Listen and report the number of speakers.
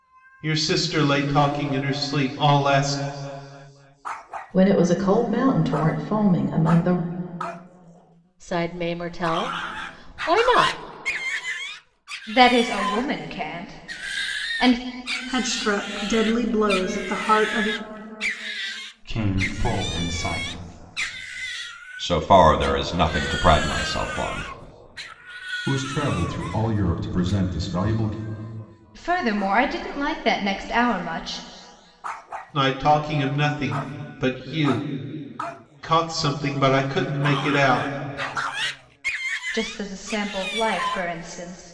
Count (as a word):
eight